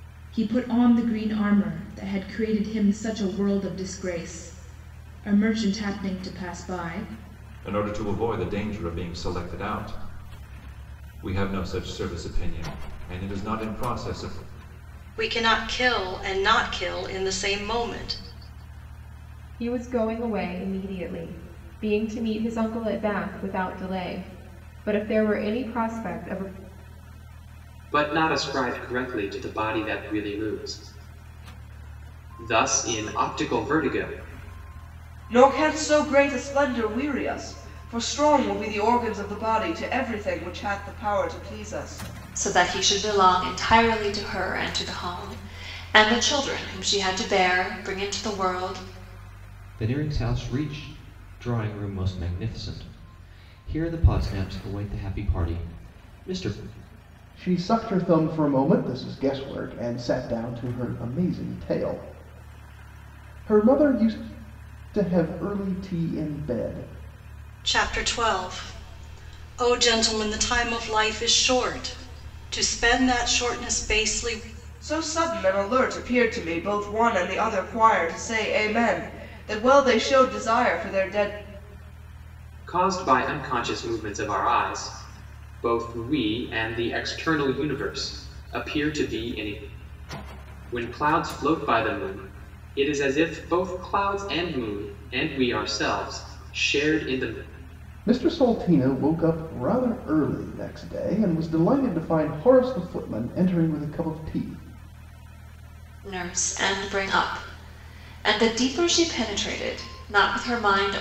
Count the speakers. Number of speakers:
nine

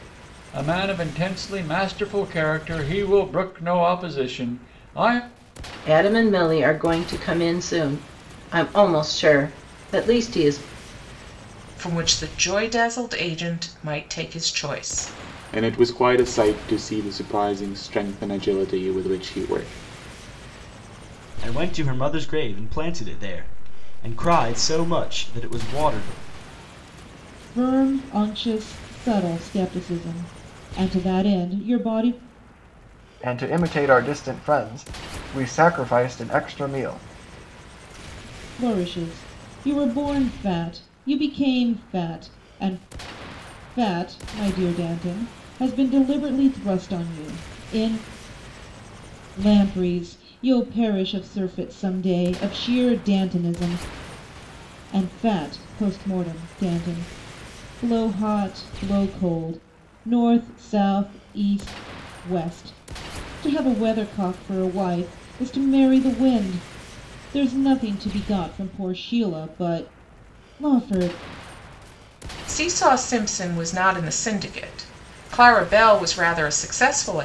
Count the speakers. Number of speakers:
seven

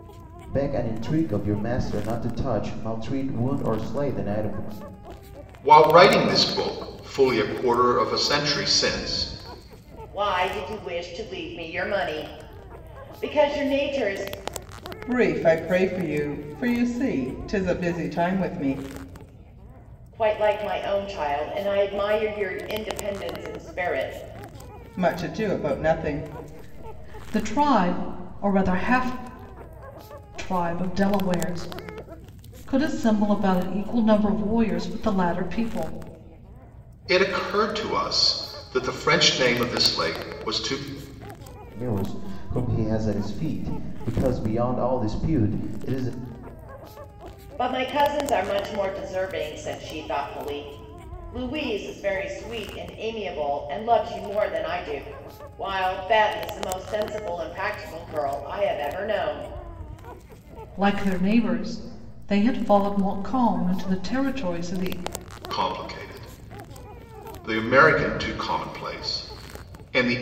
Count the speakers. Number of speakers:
four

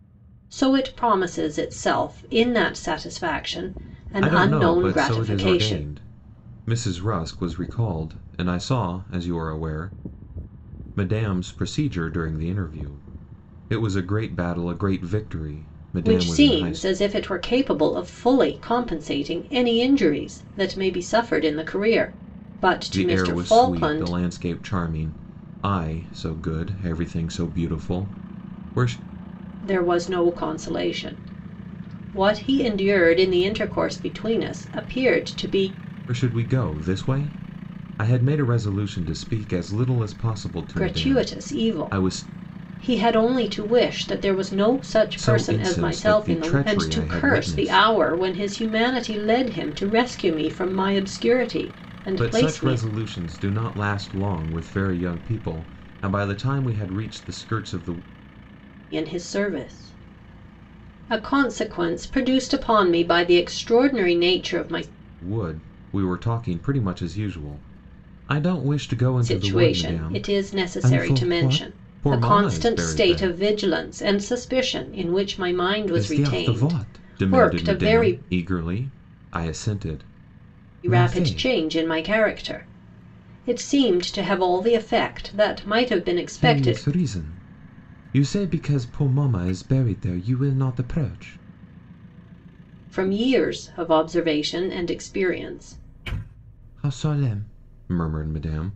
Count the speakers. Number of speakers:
two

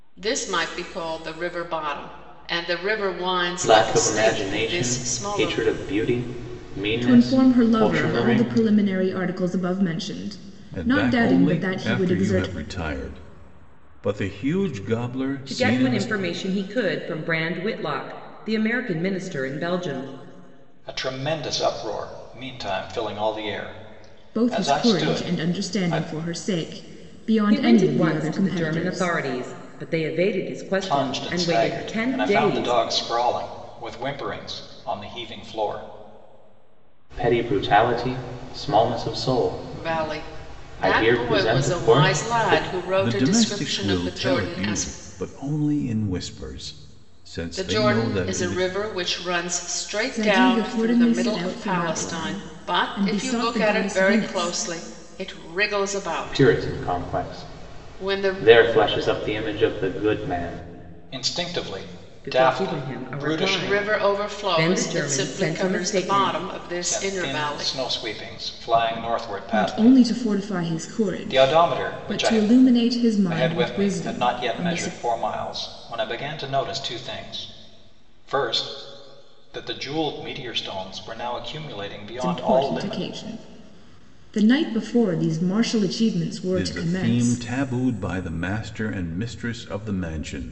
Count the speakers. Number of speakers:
six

